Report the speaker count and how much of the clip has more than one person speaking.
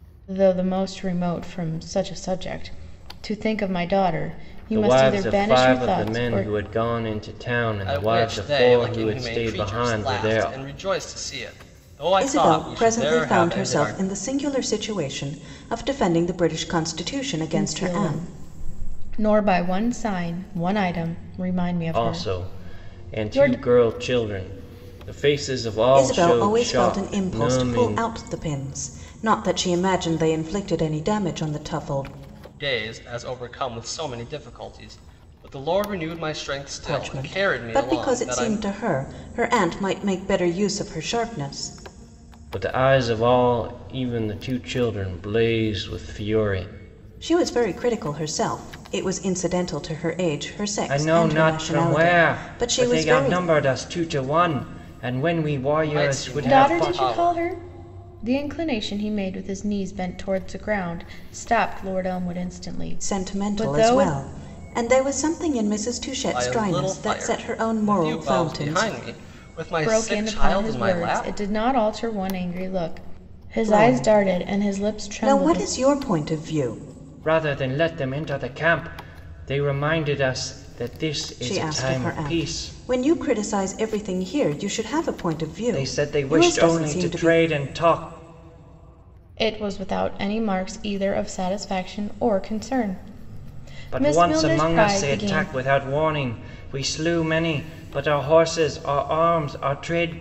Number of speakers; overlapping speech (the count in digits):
4, about 29%